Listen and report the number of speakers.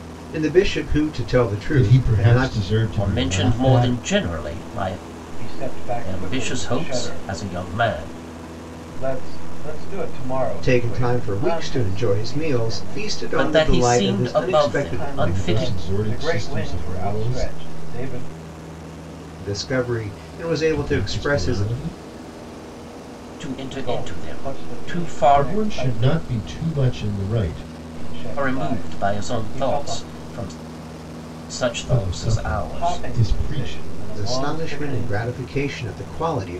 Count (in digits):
4